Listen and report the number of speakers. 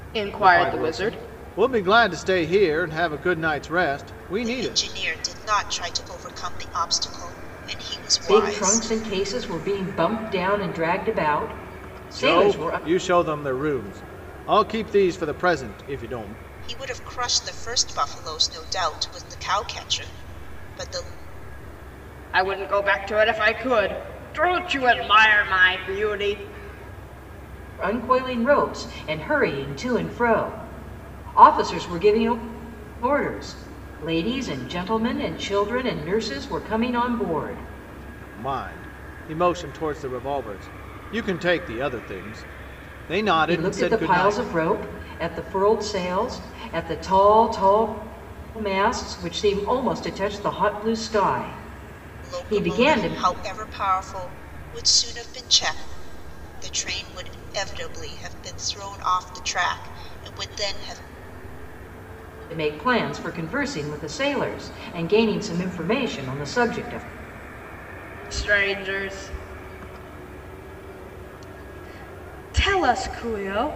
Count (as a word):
four